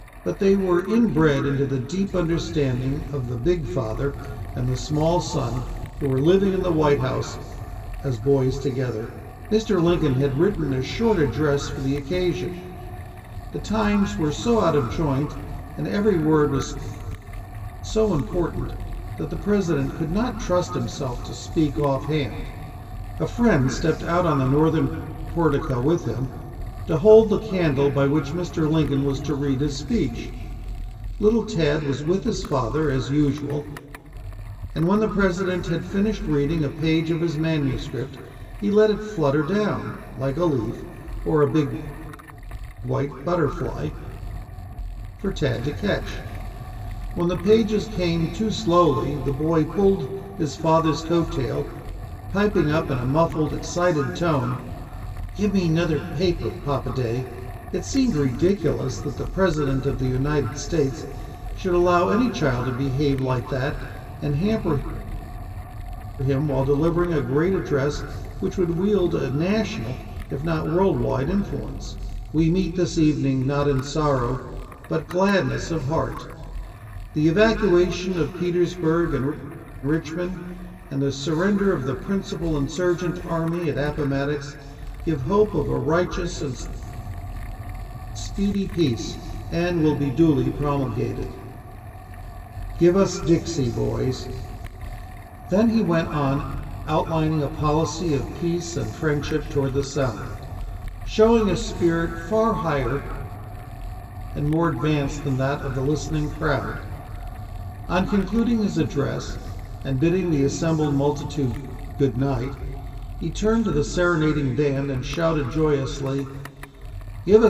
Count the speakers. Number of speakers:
1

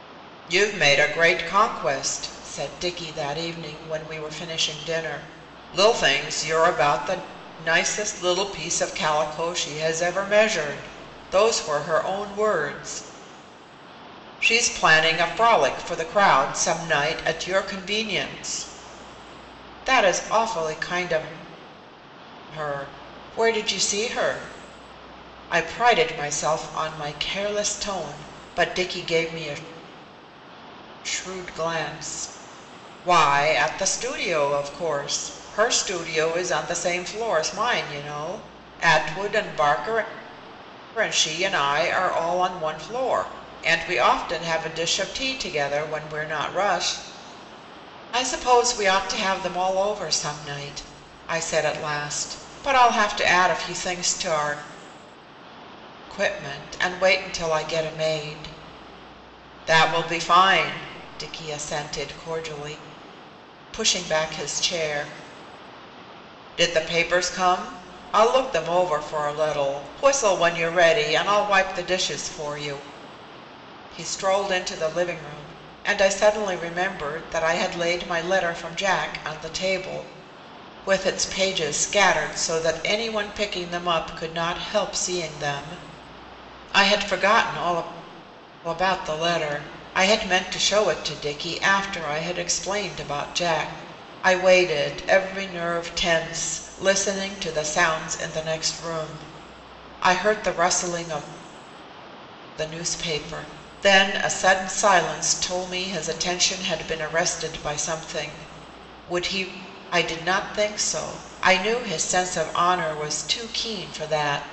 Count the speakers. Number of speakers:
1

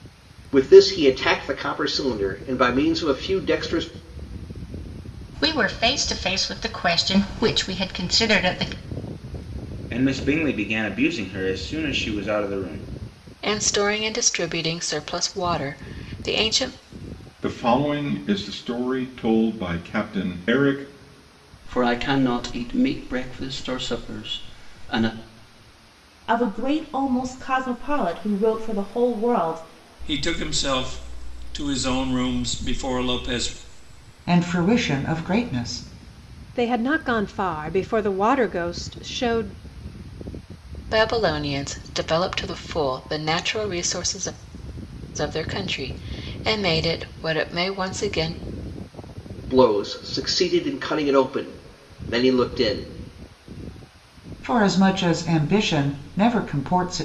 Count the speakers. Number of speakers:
10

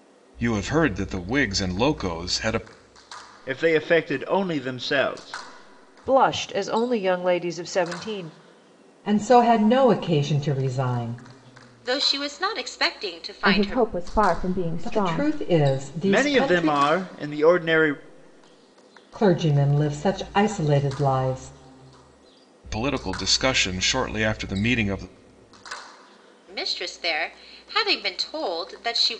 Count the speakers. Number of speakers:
6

